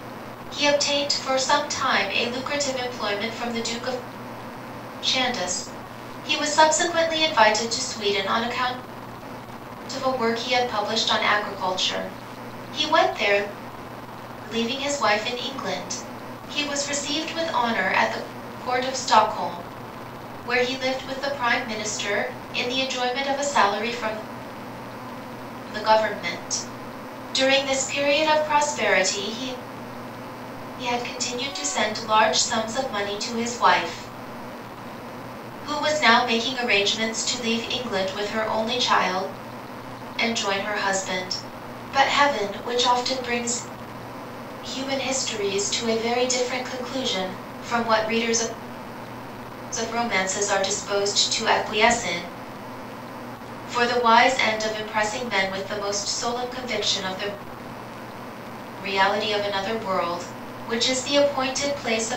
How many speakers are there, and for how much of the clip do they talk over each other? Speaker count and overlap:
1, no overlap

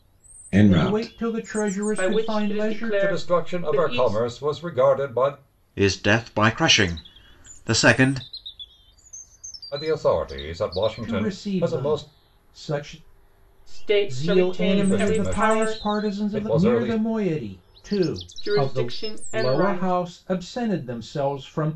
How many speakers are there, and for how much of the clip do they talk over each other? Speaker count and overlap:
5, about 37%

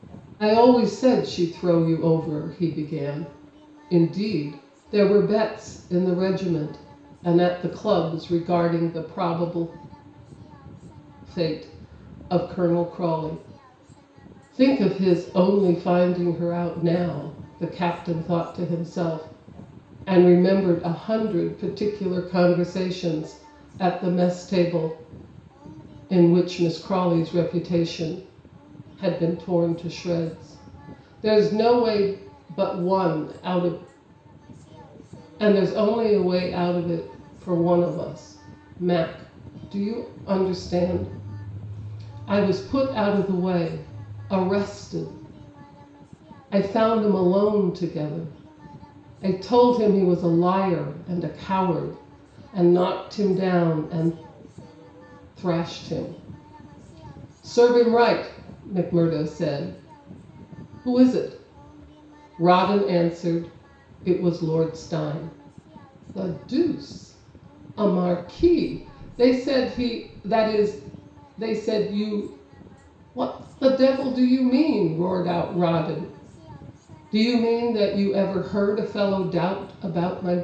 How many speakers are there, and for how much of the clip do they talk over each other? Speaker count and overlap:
1, no overlap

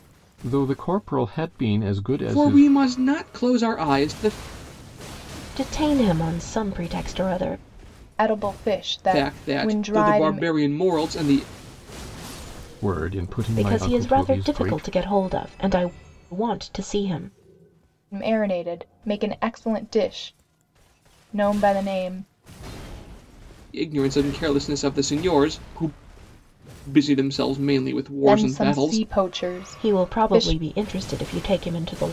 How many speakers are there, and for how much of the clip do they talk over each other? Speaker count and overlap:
4, about 16%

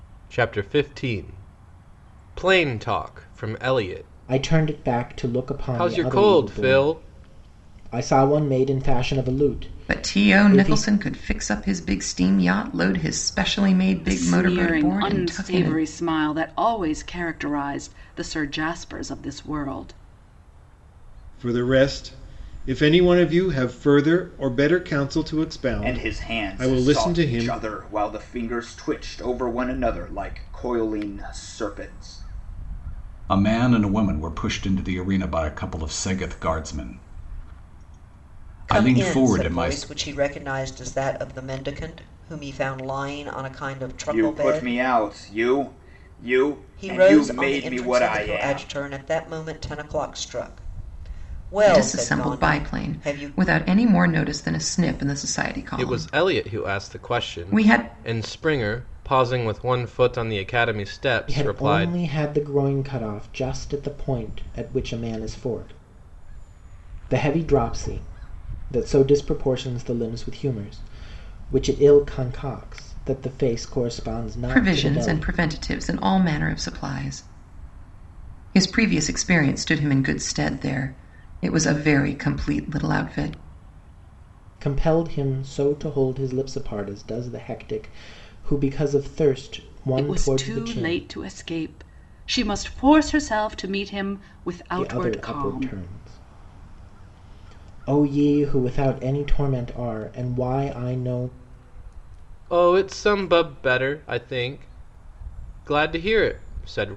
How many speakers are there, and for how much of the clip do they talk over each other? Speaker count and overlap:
8, about 18%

